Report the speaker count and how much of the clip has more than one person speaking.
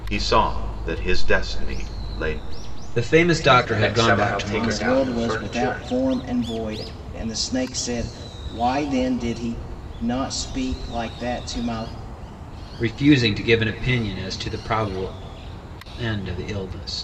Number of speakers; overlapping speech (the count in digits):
4, about 13%